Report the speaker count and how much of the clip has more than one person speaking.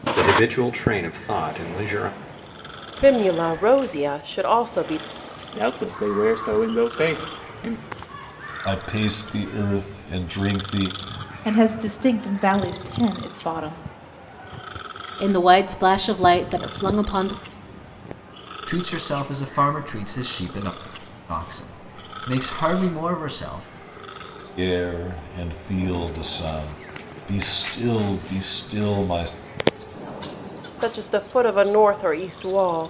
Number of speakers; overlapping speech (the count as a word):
seven, no overlap